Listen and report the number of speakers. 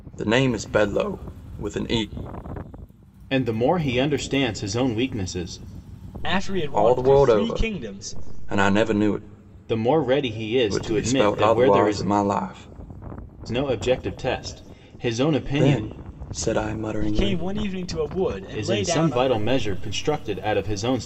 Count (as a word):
three